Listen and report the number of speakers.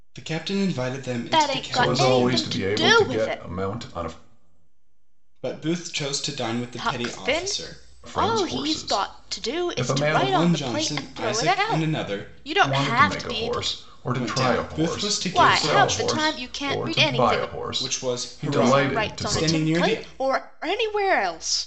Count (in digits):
3